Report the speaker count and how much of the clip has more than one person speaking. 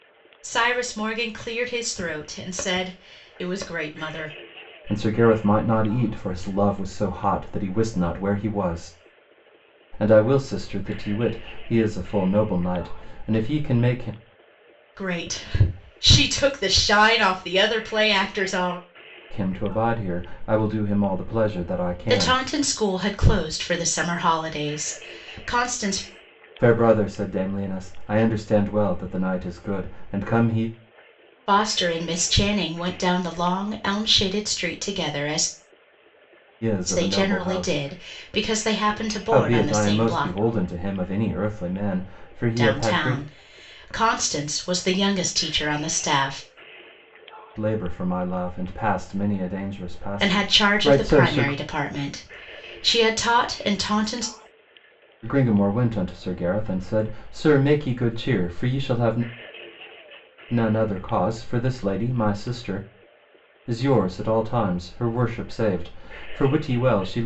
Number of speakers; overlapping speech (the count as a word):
two, about 7%